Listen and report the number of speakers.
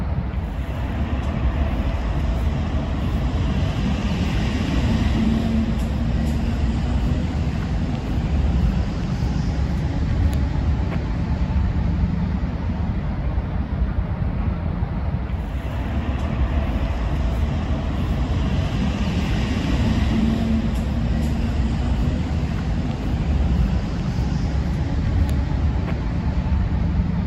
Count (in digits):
0